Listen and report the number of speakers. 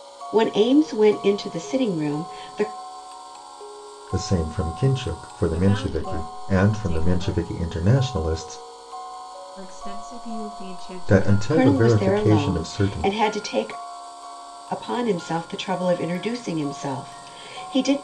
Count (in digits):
3